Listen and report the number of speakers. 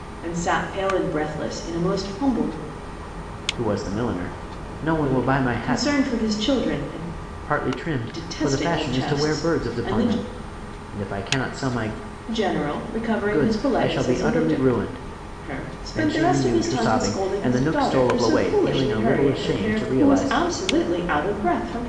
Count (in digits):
2